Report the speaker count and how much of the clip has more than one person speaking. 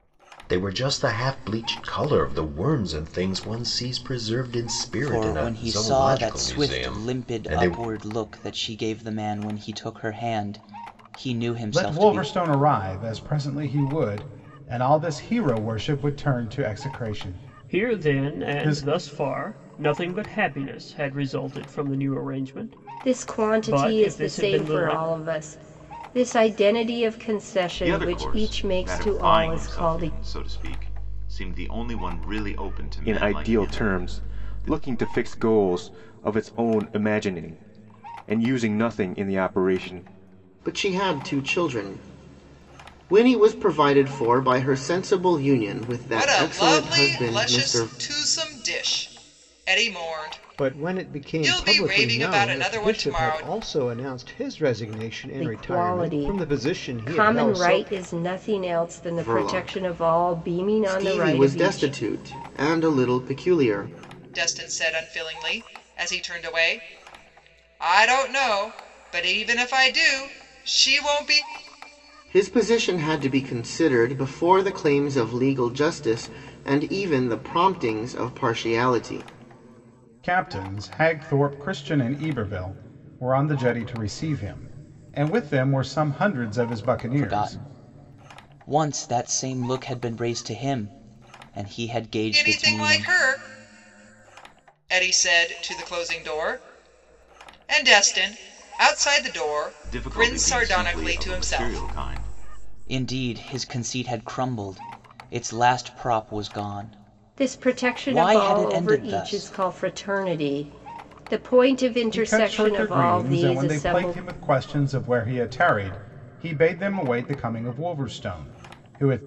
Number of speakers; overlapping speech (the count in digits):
10, about 24%